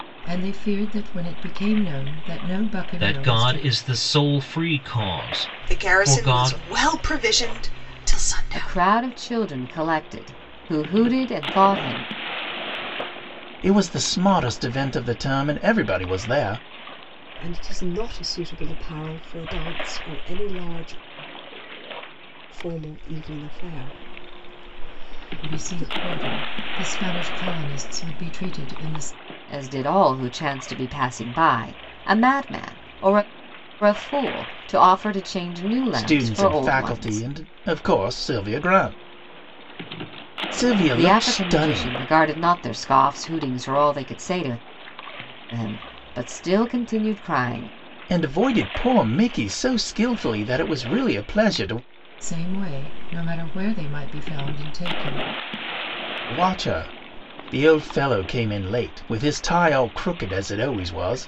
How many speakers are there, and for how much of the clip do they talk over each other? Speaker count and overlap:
six, about 8%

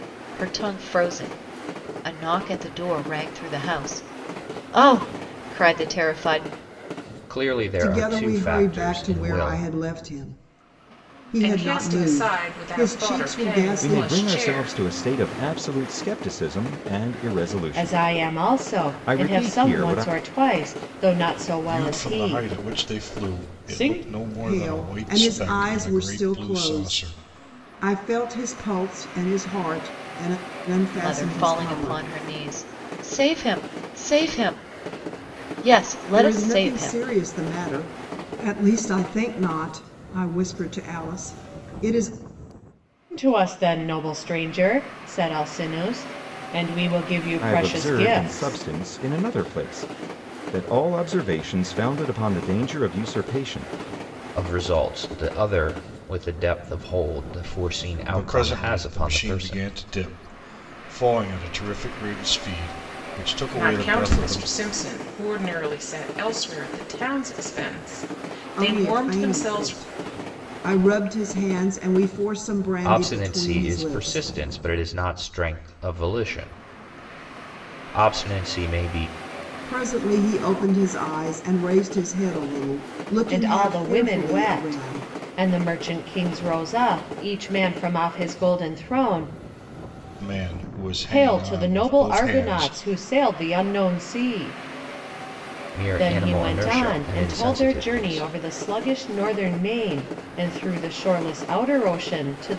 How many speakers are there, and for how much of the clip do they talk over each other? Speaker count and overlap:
seven, about 27%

